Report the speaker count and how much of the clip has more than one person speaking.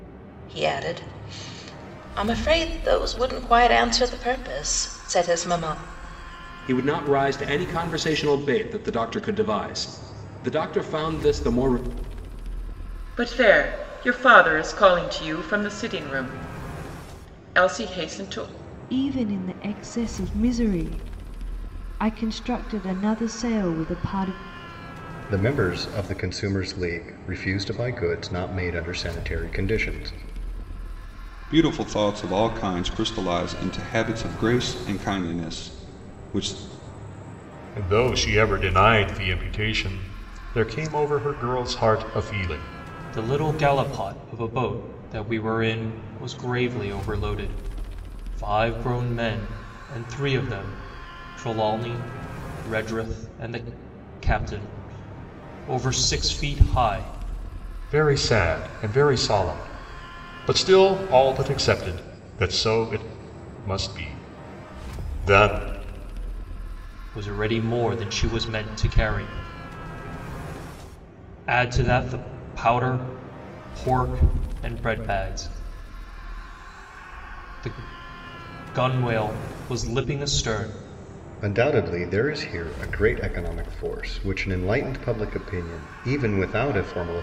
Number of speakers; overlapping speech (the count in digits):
8, no overlap